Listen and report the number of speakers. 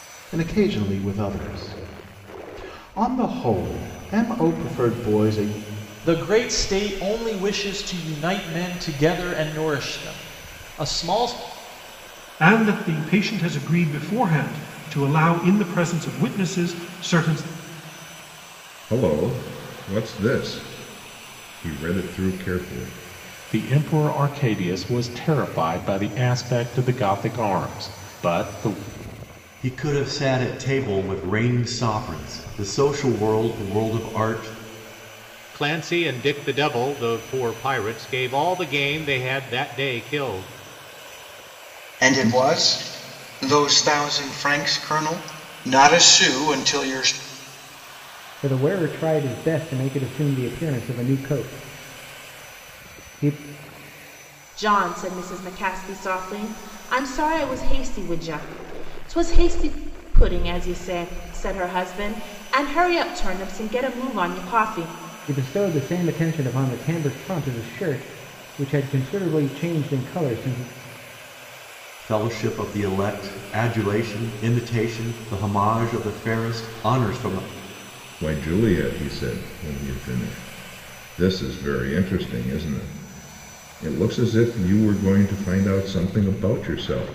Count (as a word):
ten